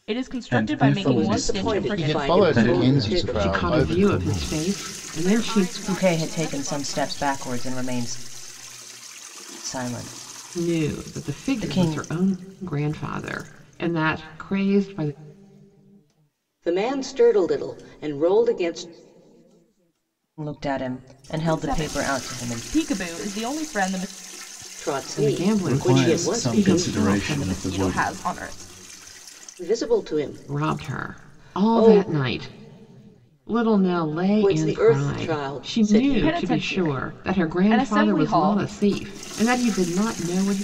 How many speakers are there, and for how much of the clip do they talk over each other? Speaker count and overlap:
eight, about 43%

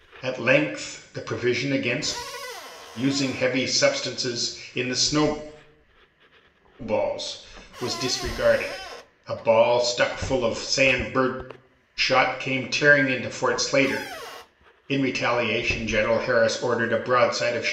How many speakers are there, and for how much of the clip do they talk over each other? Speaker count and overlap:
one, no overlap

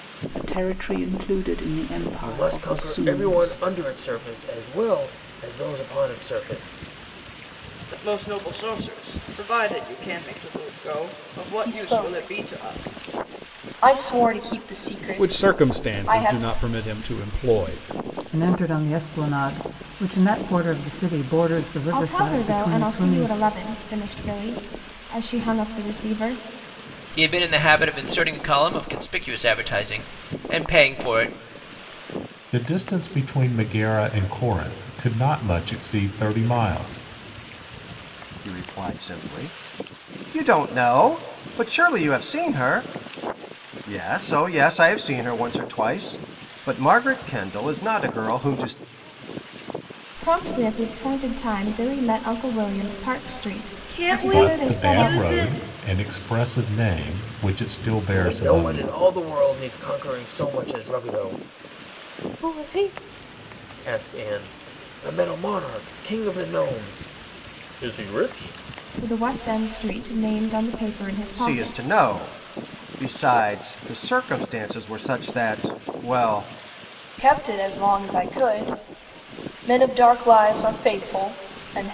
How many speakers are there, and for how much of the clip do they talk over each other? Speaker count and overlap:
ten, about 11%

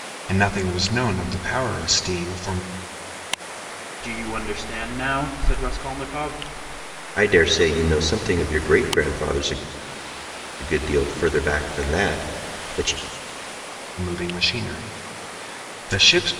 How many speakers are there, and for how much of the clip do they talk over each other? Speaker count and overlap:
three, no overlap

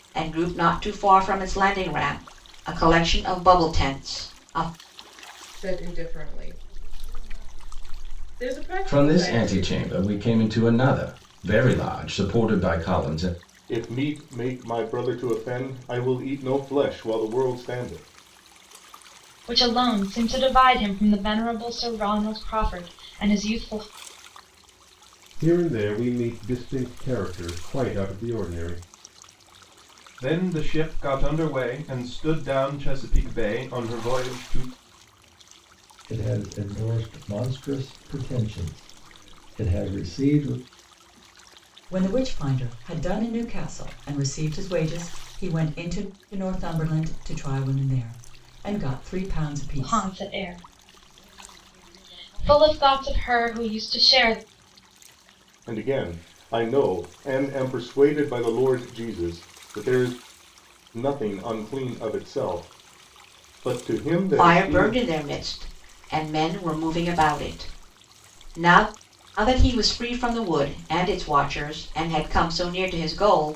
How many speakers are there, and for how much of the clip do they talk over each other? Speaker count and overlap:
nine, about 3%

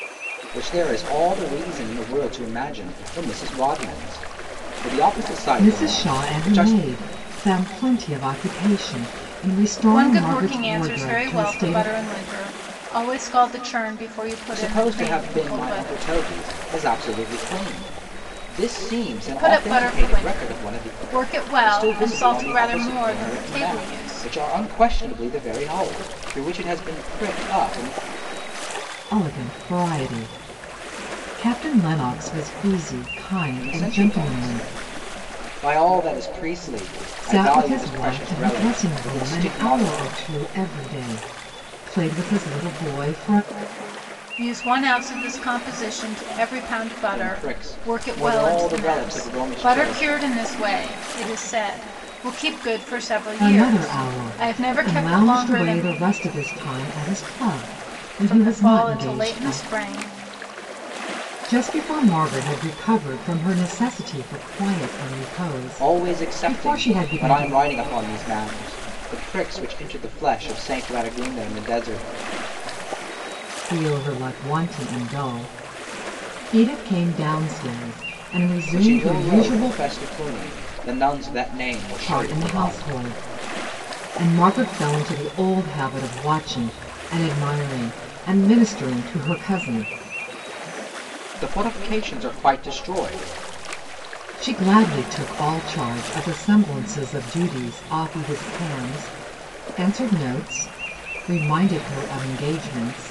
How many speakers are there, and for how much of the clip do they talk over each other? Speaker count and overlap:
three, about 23%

